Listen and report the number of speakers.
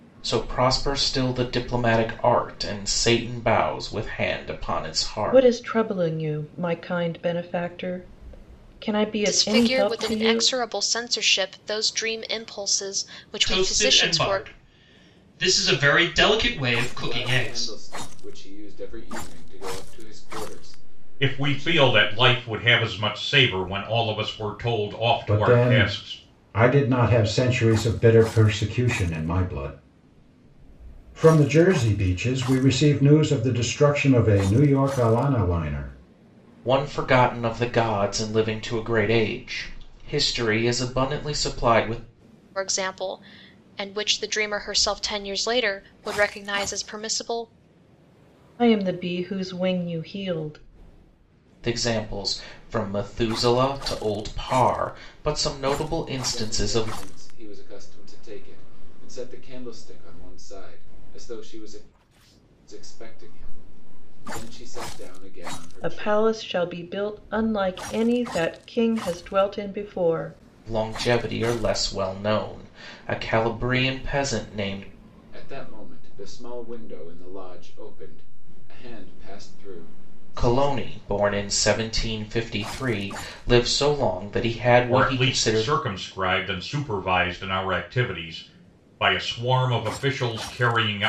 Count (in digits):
7